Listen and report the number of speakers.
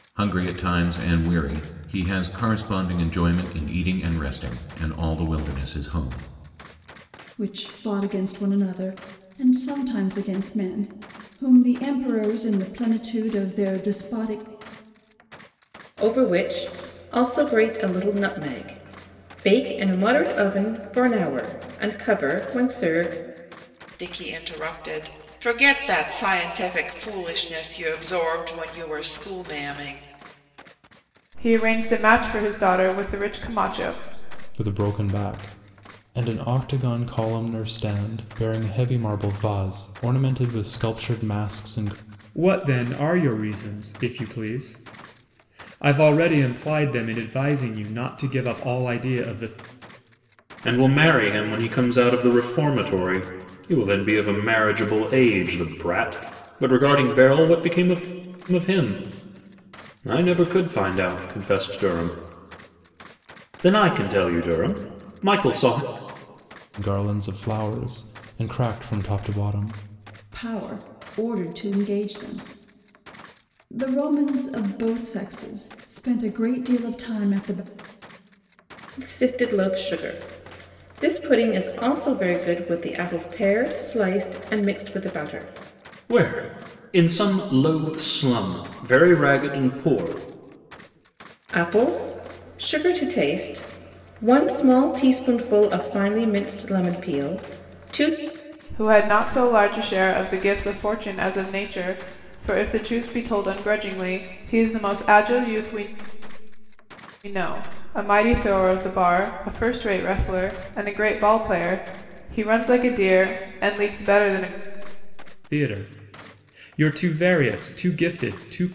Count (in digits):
8